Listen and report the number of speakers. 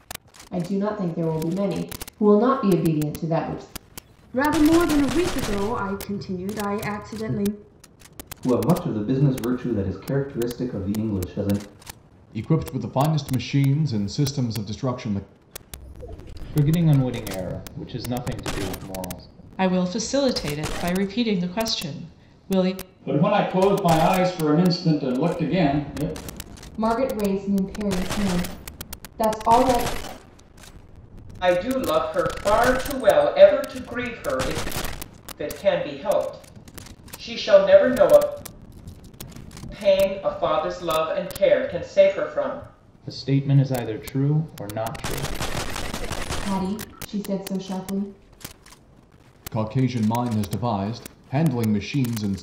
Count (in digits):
9